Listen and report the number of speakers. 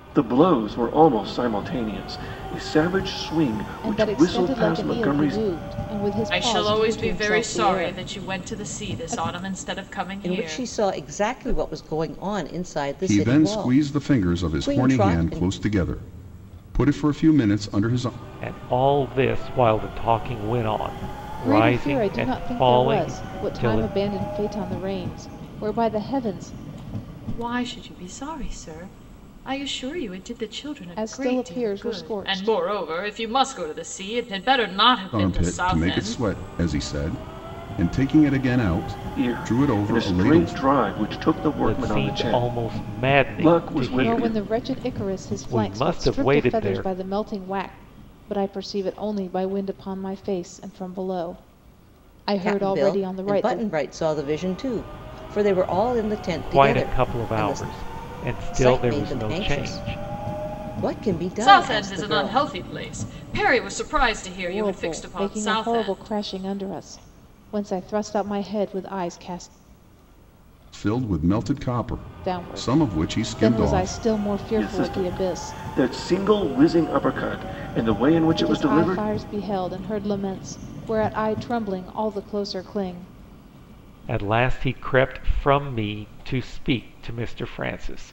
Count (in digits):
6